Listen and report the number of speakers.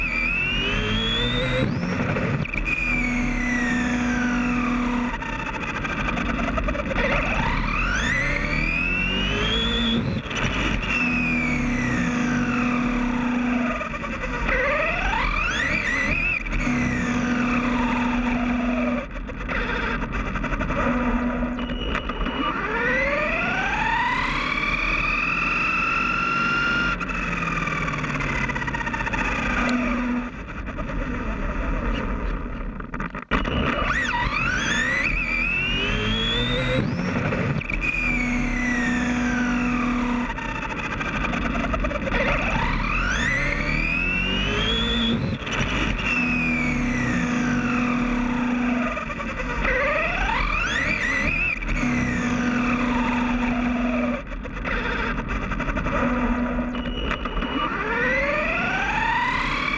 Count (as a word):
zero